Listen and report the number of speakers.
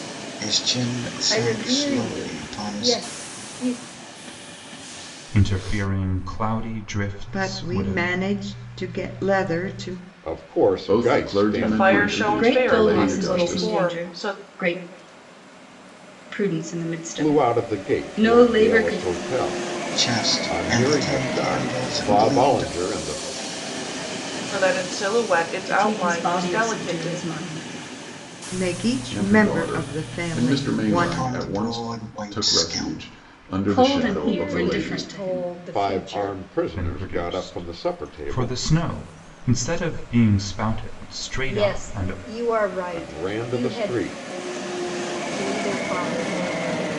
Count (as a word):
eight